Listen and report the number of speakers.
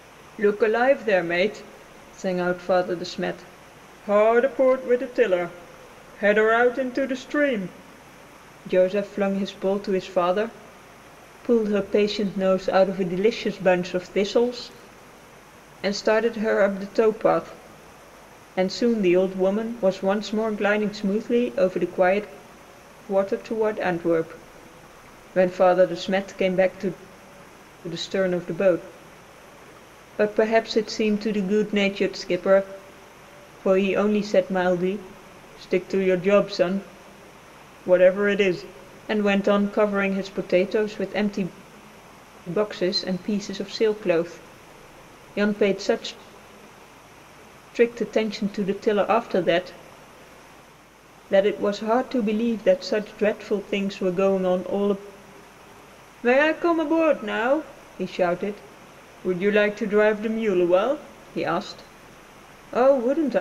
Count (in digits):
1